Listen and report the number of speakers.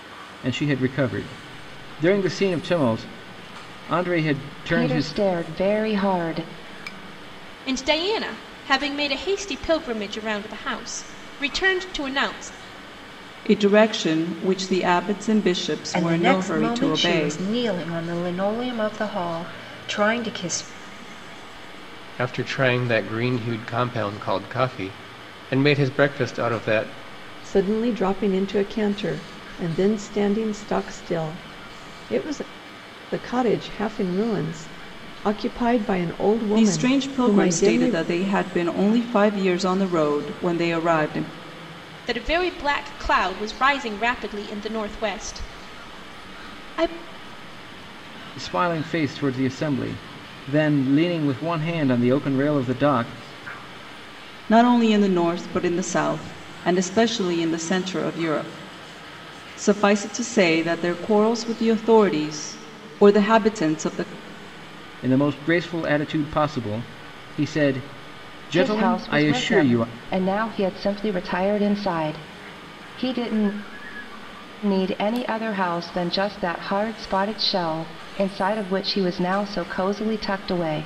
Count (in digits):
7